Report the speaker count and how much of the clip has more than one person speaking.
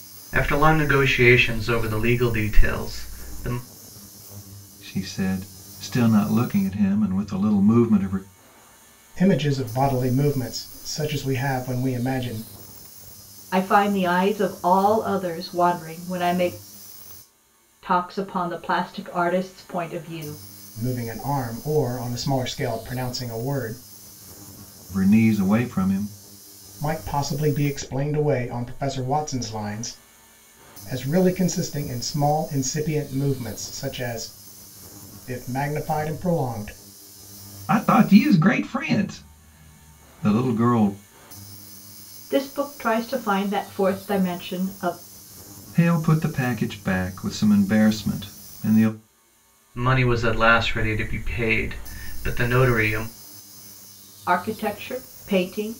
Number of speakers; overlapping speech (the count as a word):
four, no overlap